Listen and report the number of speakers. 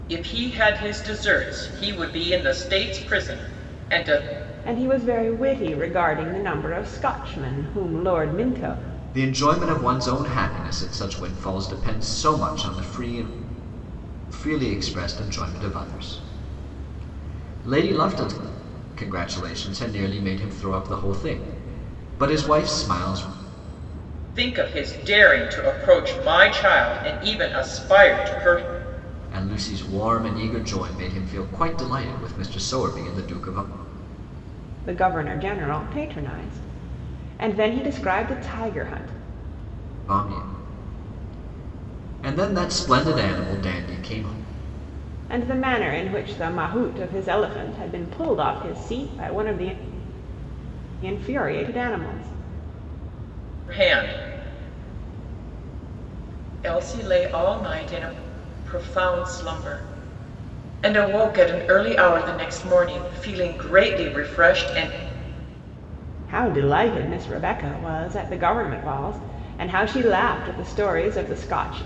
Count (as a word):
three